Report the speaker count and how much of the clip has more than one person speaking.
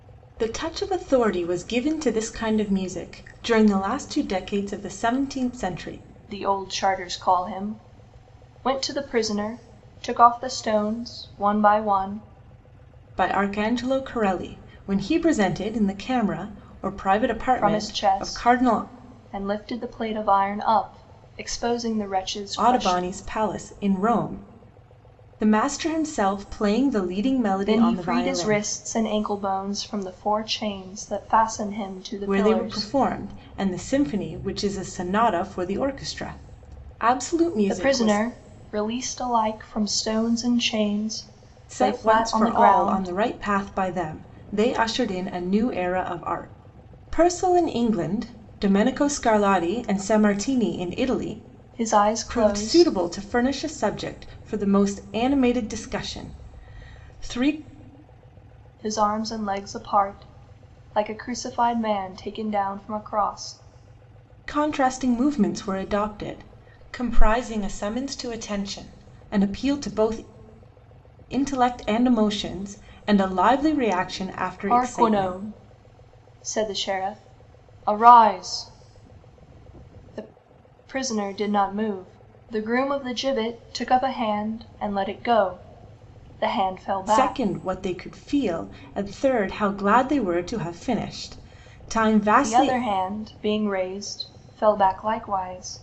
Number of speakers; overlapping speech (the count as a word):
two, about 9%